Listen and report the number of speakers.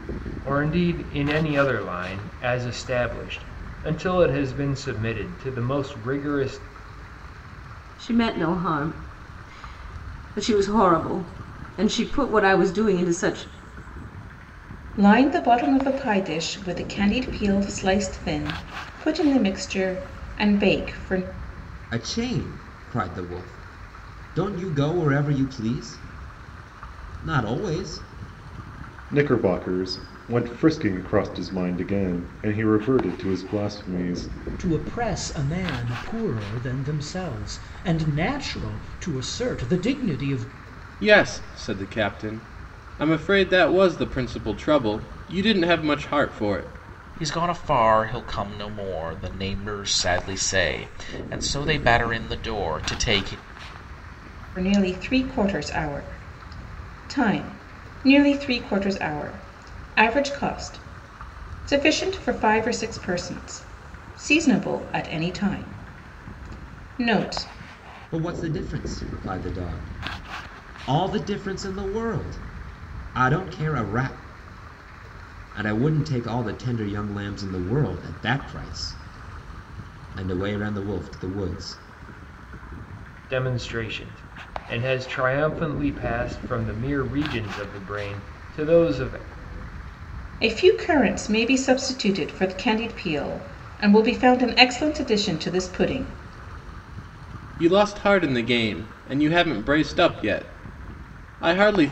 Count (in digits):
8